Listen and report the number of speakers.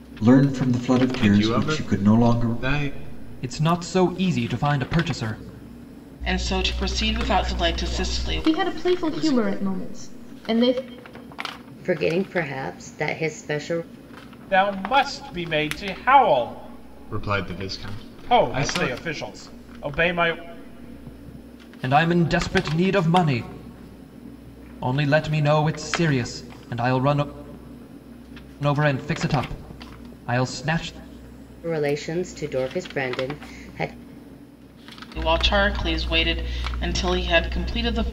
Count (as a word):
eight